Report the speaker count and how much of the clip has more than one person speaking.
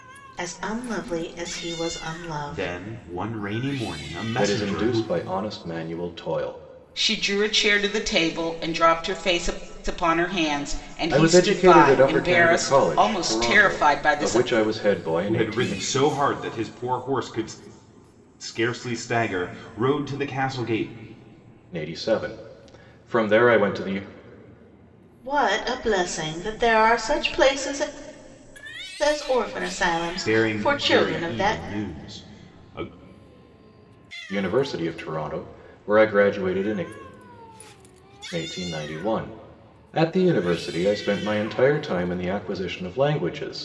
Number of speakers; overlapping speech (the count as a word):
four, about 15%